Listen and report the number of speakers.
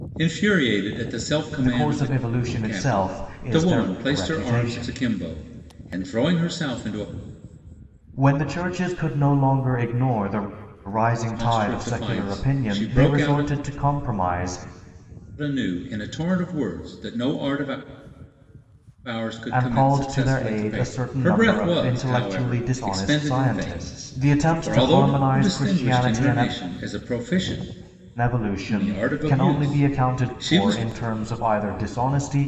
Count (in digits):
2